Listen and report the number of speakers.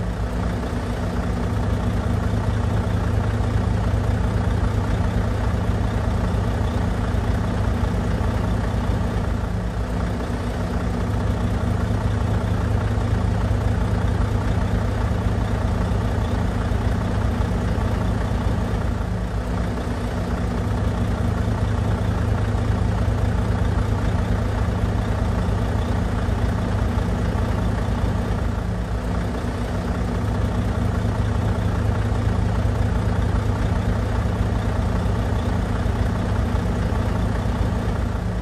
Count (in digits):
0